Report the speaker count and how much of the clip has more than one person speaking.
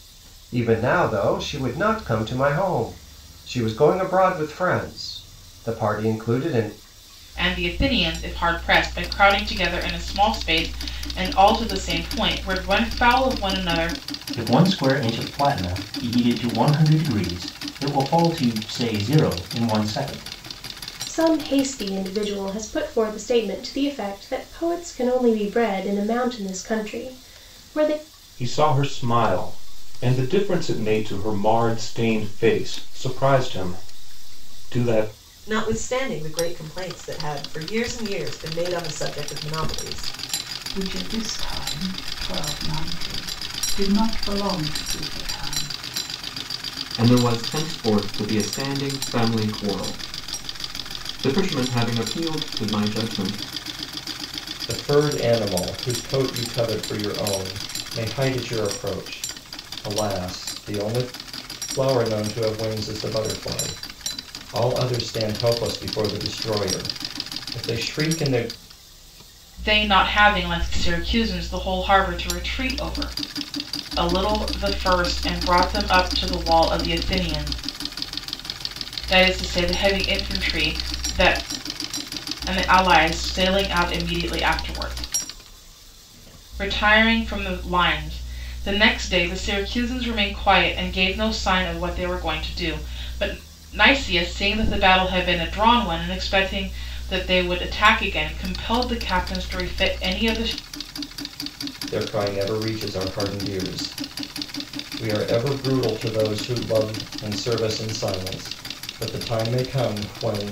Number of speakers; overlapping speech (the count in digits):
9, no overlap